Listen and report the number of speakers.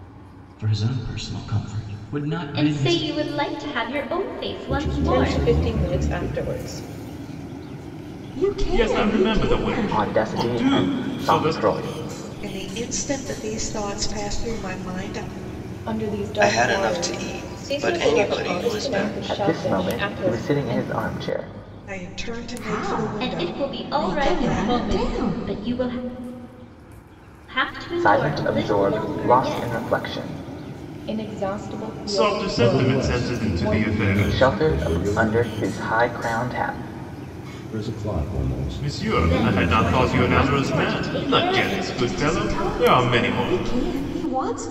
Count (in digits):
10